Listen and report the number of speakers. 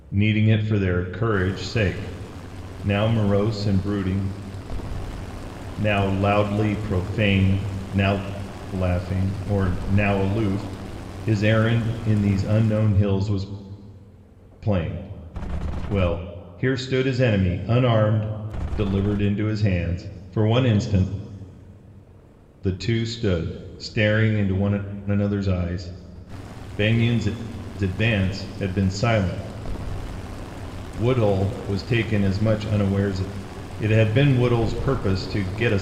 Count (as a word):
one